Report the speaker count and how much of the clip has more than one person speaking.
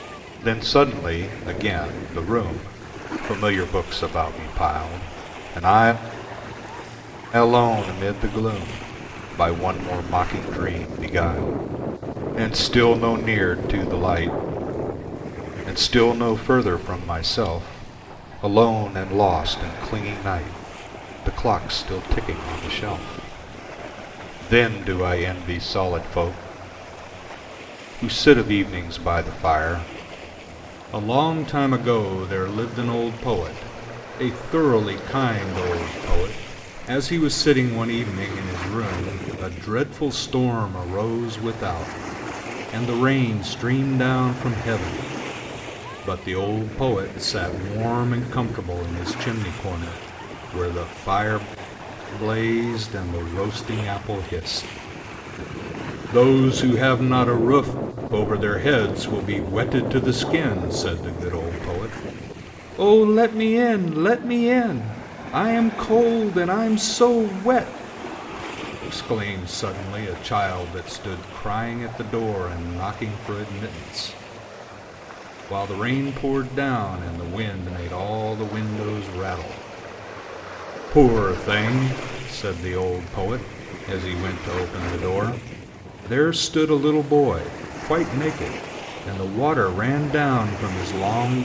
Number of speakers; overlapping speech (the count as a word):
one, no overlap